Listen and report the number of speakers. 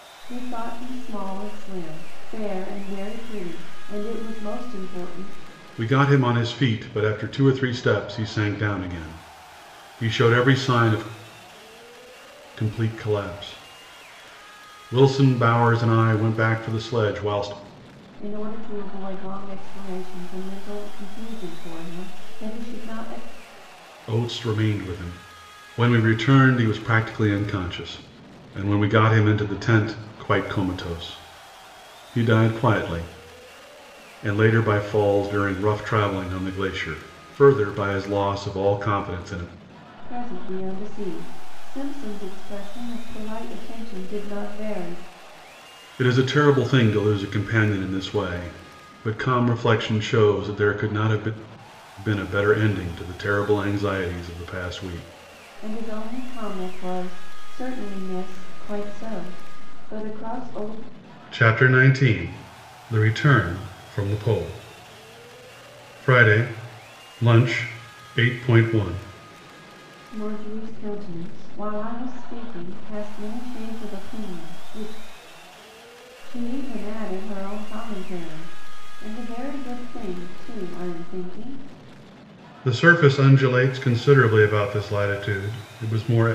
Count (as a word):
two